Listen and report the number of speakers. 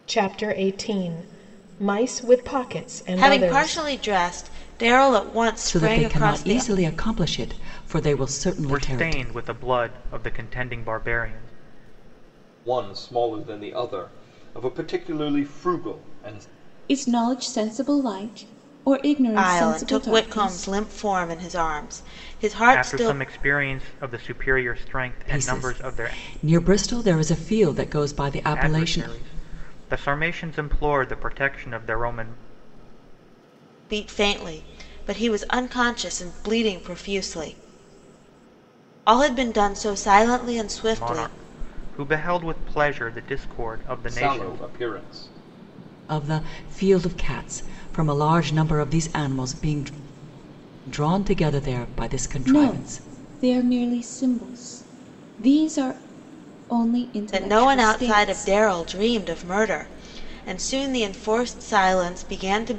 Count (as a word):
six